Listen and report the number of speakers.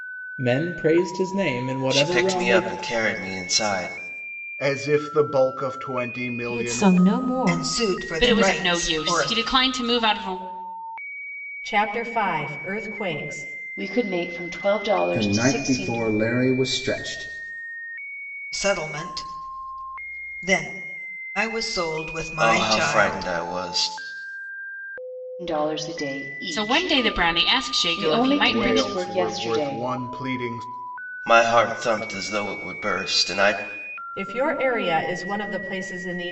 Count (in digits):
9